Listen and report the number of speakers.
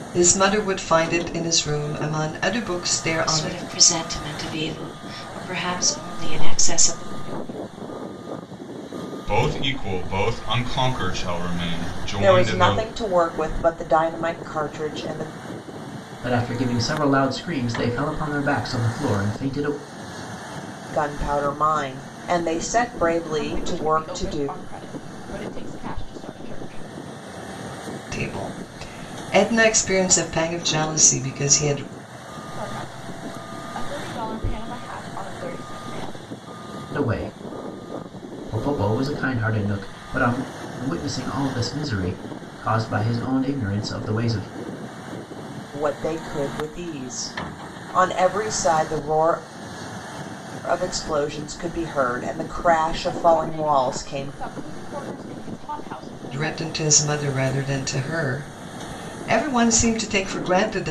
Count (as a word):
six